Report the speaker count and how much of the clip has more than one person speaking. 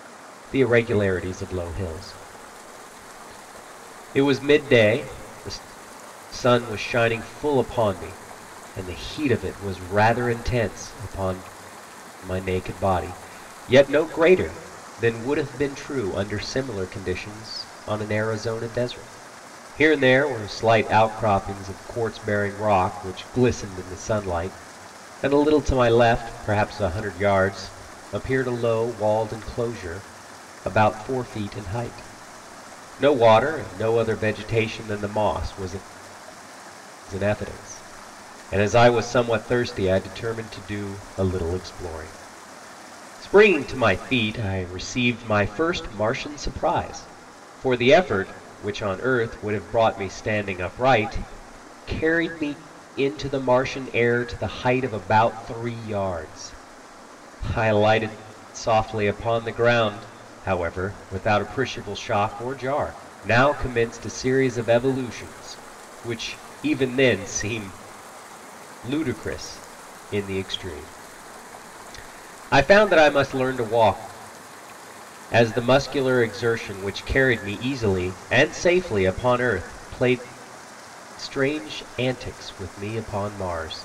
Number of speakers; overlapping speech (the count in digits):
1, no overlap